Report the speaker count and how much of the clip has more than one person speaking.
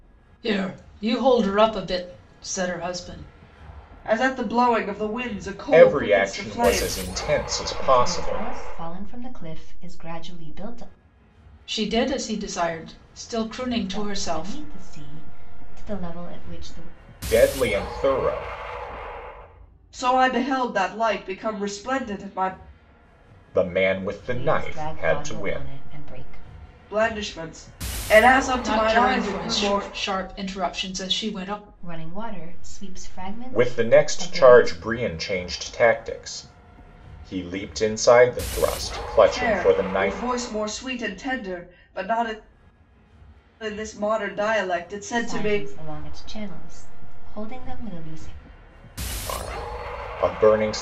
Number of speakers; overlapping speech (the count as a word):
four, about 16%